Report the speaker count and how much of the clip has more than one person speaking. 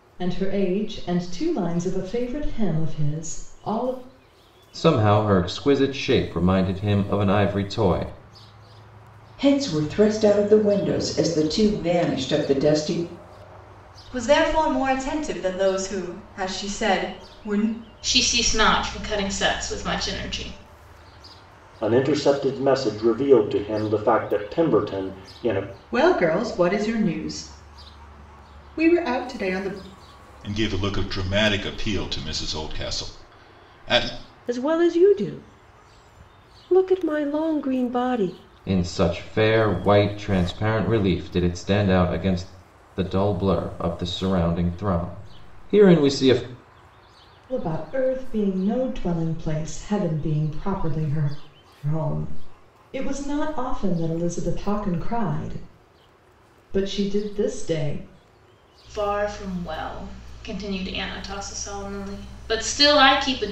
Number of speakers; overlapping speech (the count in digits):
9, no overlap